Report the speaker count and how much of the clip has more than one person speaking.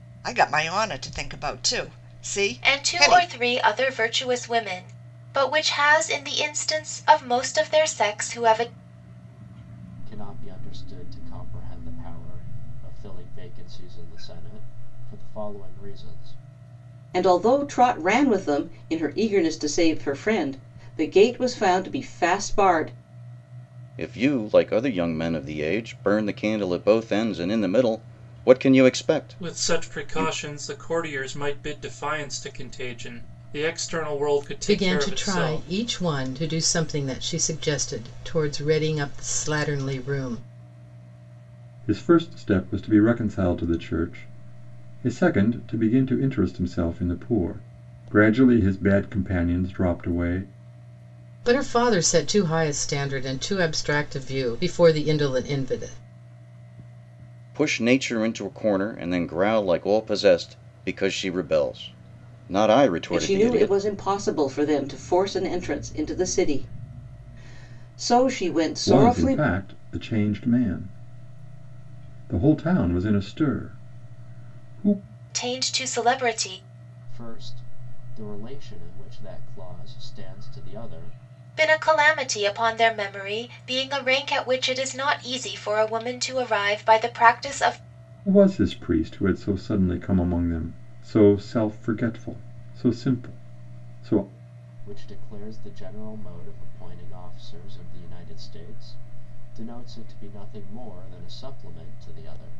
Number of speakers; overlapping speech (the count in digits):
8, about 4%